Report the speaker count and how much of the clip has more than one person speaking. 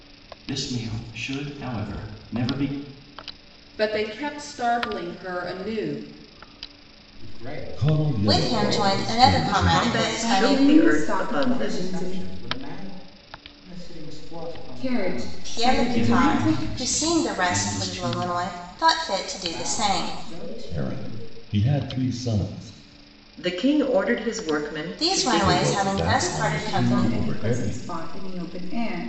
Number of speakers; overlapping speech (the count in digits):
7, about 42%